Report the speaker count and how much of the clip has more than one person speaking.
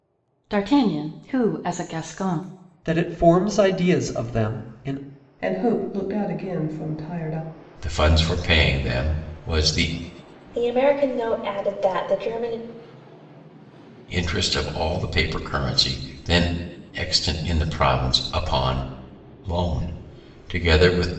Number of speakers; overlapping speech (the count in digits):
5, no overlap